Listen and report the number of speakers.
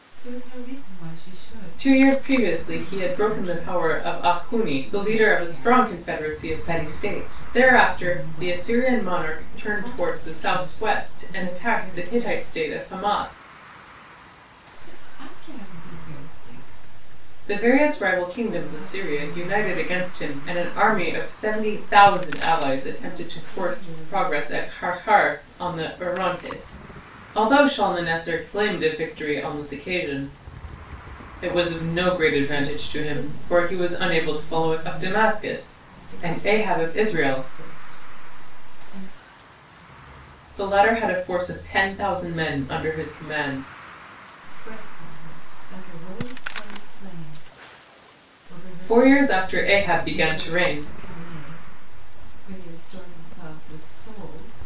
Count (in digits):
2